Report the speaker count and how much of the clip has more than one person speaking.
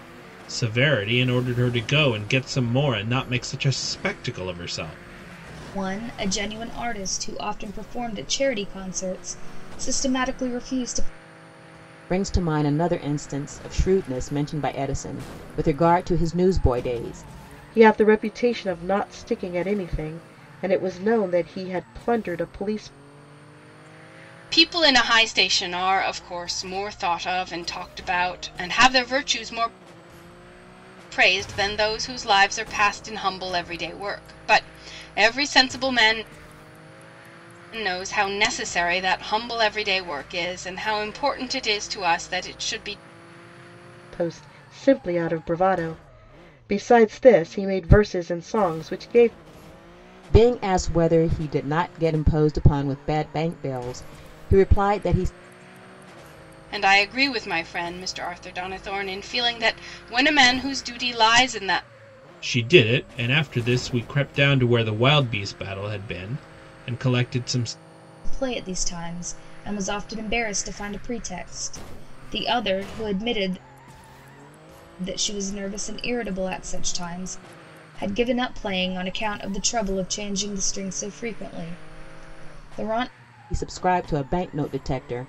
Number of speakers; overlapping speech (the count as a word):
five, no overlap